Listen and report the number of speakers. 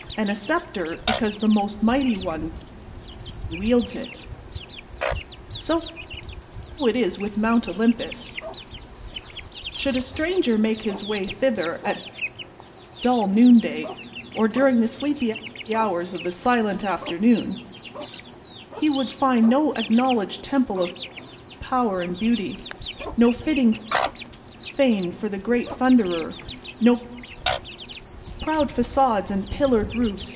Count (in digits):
1